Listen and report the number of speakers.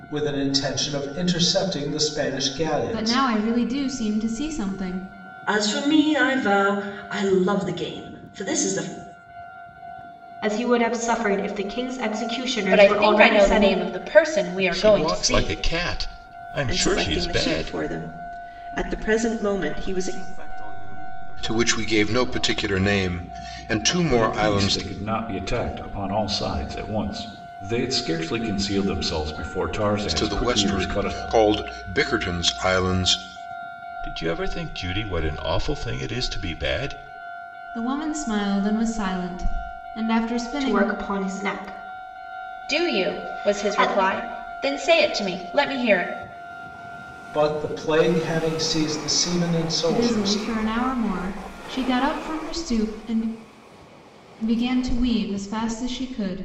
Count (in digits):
10